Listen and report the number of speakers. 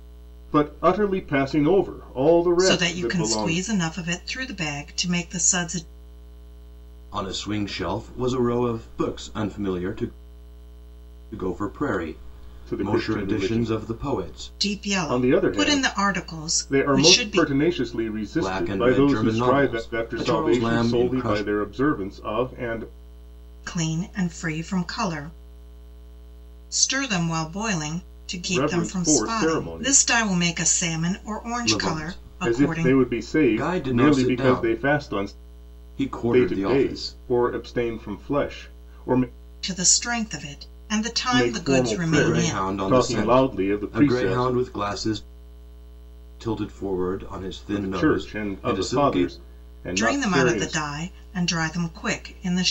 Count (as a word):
three